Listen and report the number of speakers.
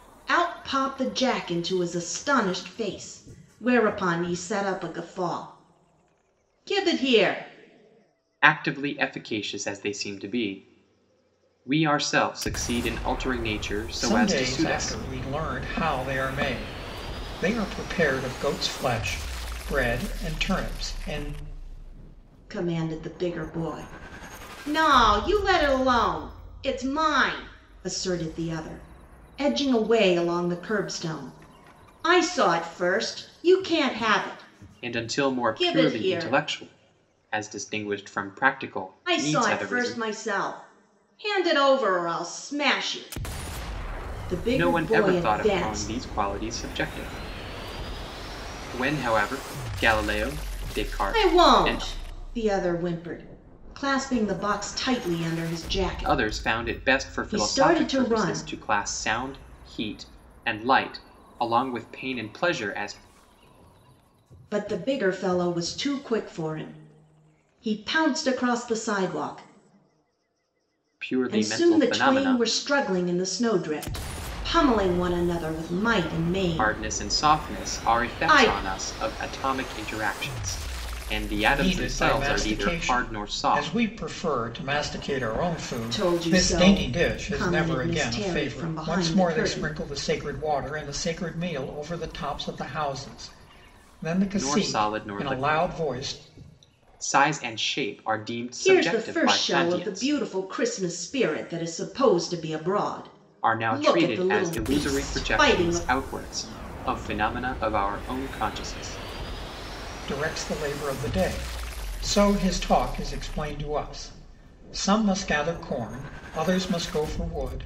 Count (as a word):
three